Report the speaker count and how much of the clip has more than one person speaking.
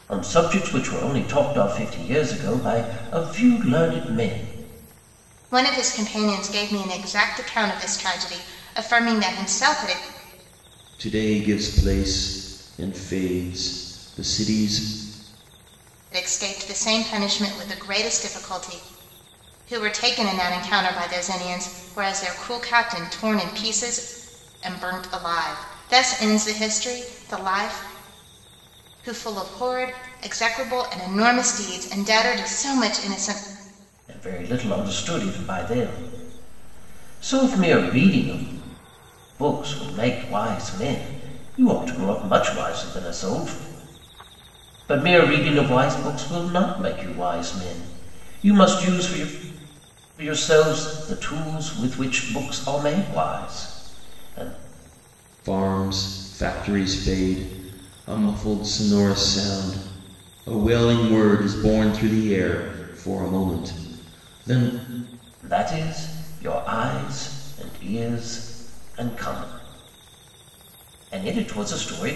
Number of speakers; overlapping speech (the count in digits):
3, no overlap